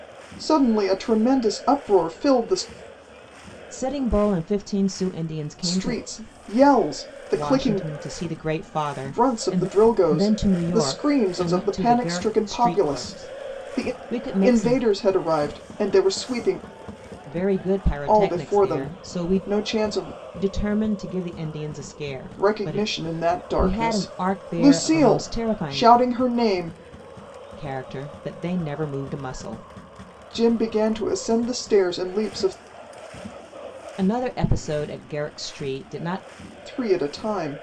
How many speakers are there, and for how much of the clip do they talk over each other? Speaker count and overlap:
two, about 25%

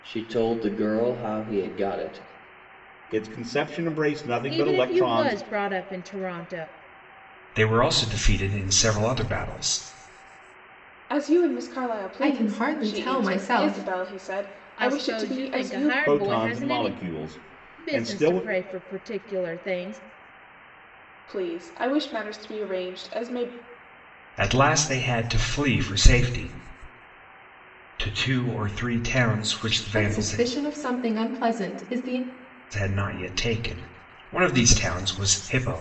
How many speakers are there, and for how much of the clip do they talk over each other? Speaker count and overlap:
six, about 17%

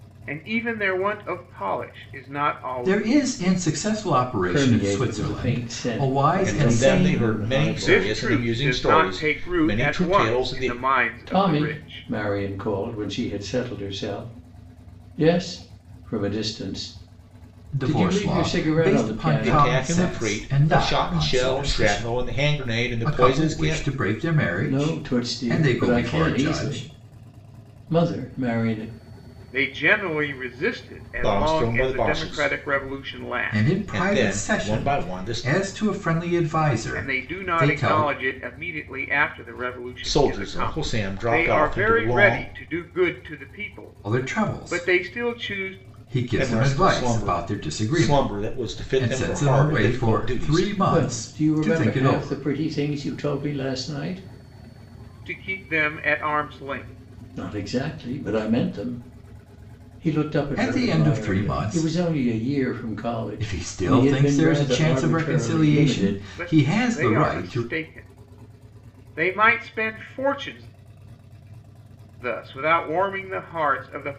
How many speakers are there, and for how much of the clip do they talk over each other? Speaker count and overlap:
four, about 49%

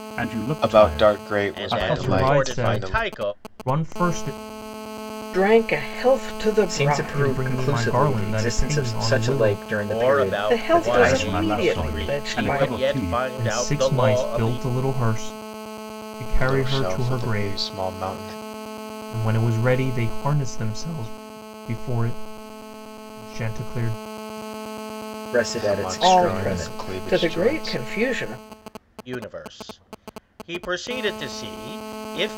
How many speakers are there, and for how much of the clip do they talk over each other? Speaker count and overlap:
six, about 43%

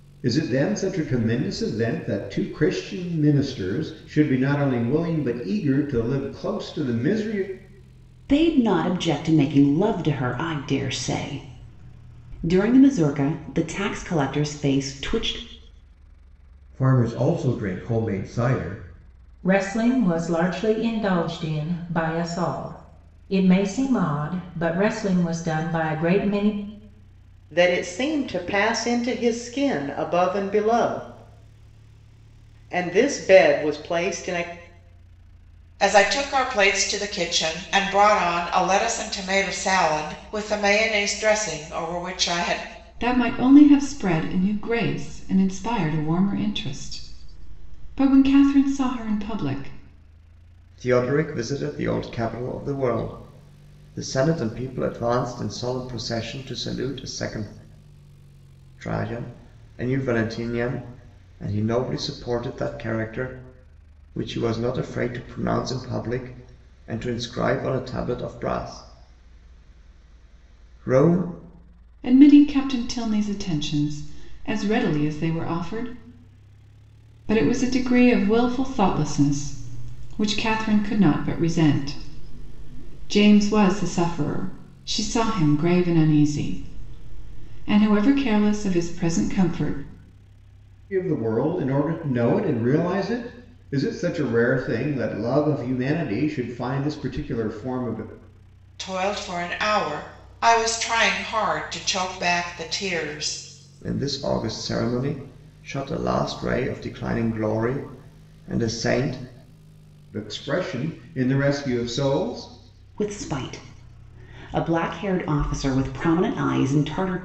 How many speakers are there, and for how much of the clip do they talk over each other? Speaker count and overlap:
eight, no overlap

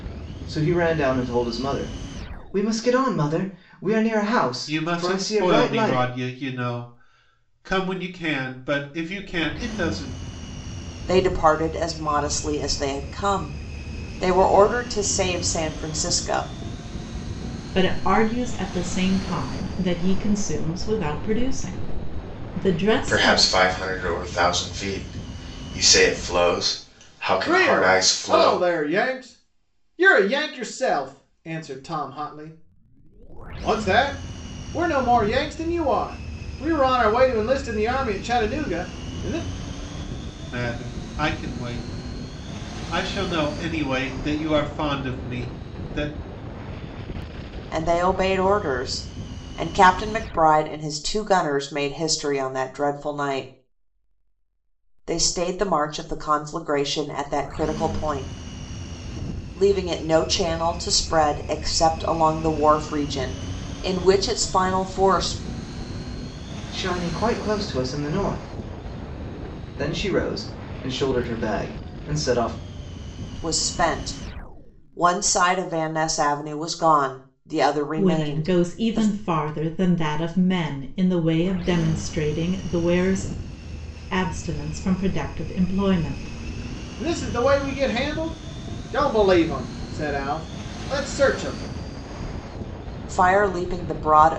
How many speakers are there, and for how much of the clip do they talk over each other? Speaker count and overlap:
six, about 5%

